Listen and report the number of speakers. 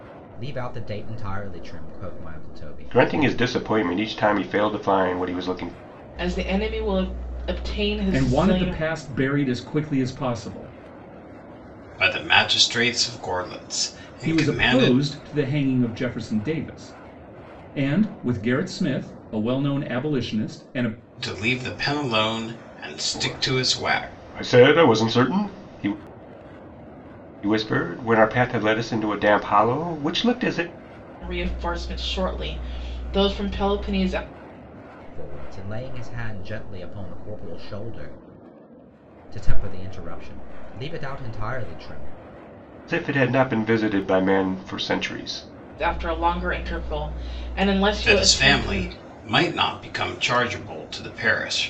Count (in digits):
5